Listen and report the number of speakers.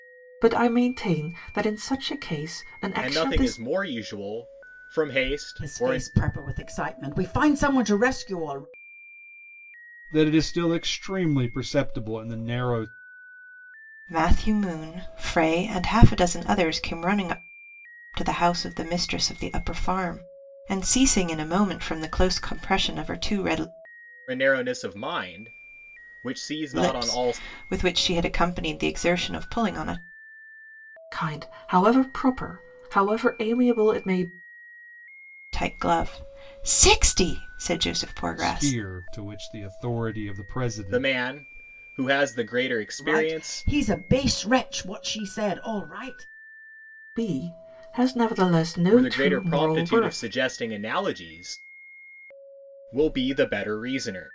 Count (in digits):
5